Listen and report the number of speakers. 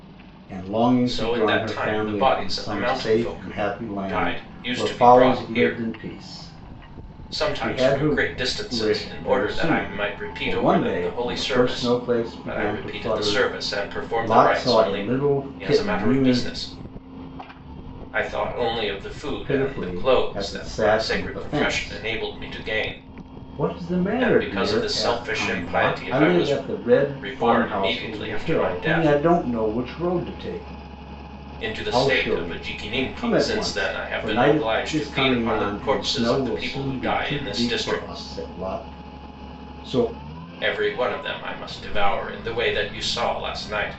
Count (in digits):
2